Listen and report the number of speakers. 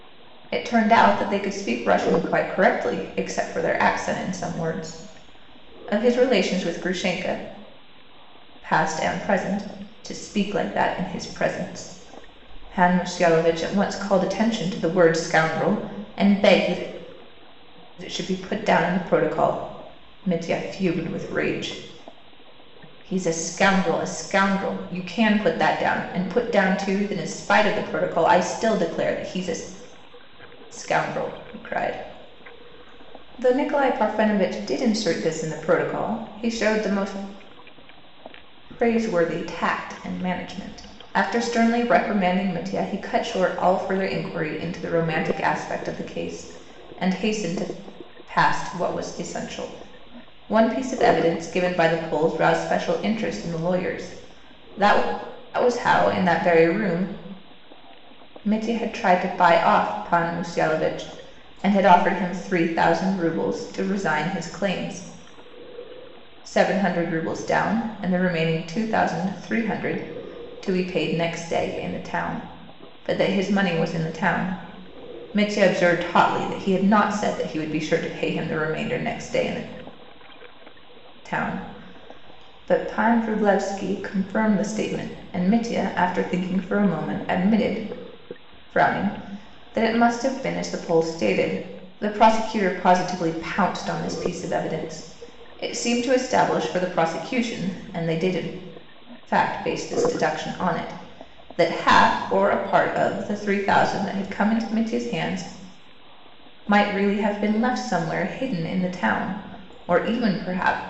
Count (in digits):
1